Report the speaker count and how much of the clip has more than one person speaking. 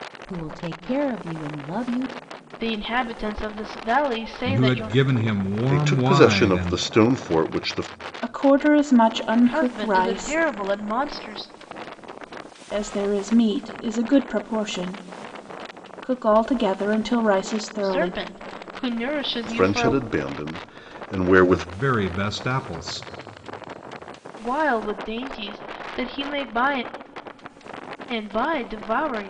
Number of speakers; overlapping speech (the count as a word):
five, about 14%